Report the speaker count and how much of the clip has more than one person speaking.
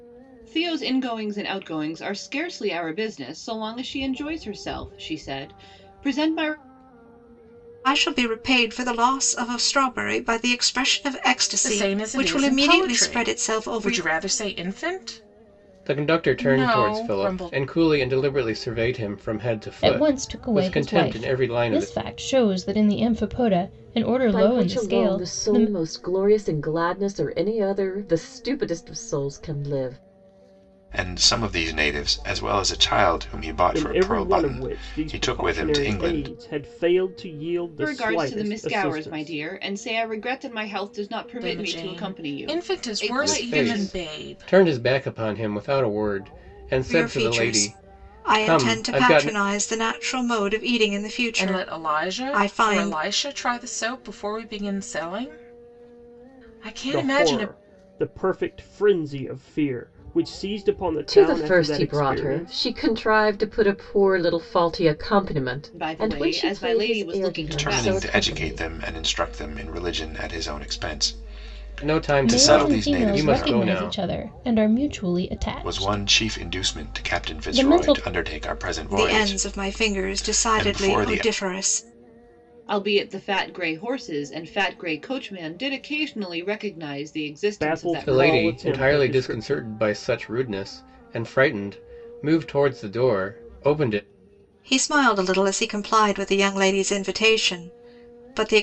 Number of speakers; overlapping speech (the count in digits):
8, about 34%